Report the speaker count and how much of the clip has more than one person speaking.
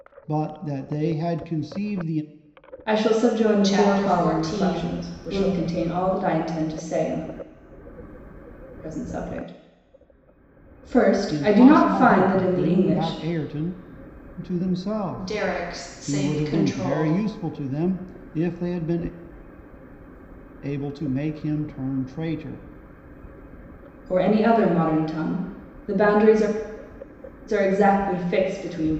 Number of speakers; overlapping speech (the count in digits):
3, about 20%